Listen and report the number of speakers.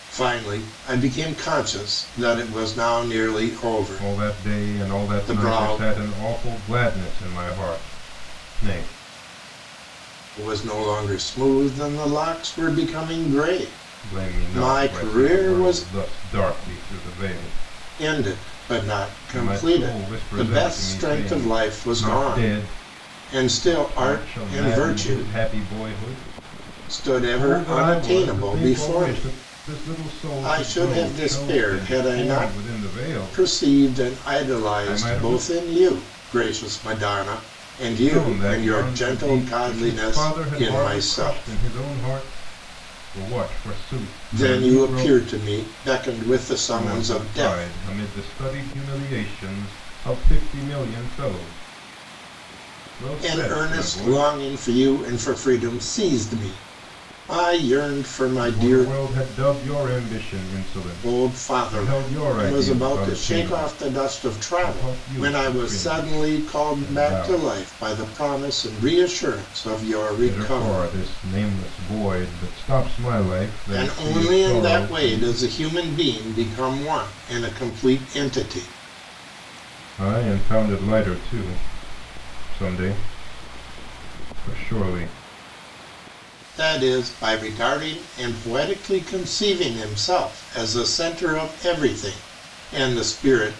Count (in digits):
2